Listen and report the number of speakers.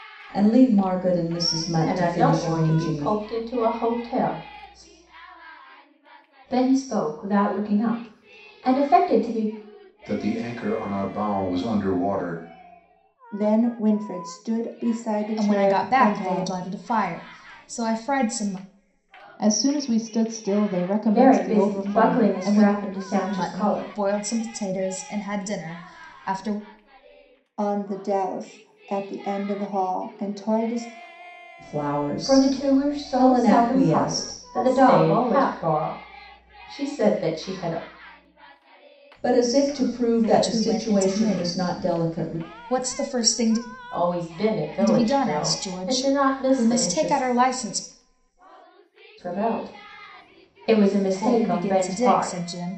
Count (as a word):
seven